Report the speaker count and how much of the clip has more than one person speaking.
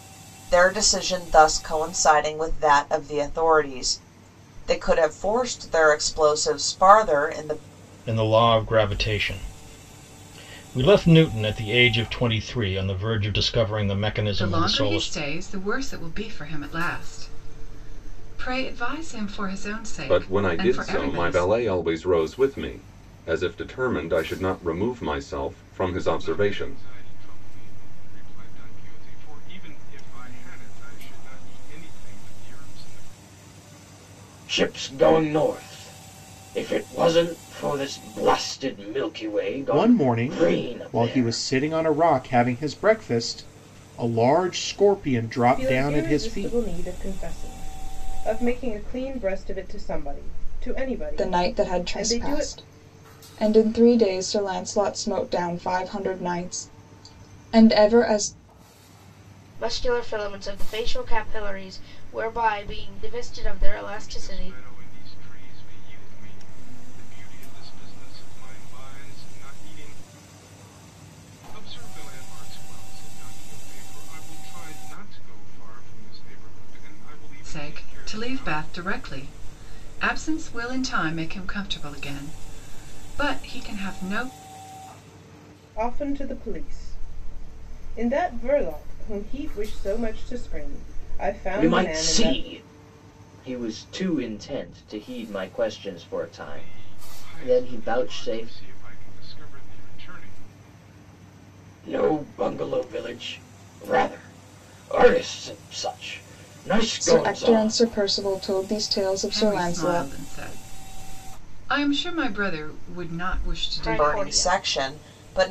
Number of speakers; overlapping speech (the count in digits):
10, about 14%